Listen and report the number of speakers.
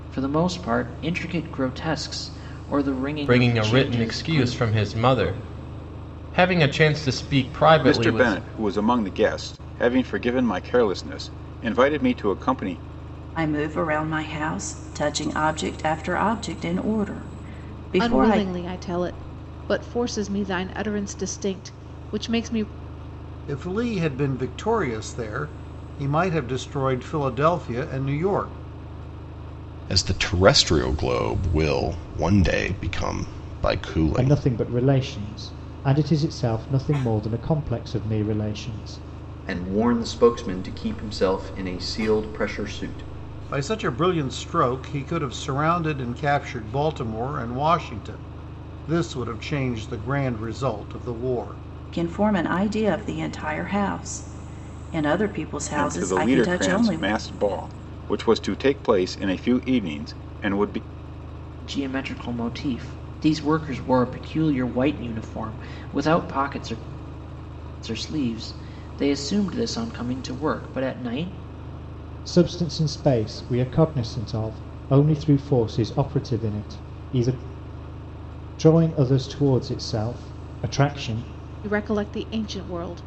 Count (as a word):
nine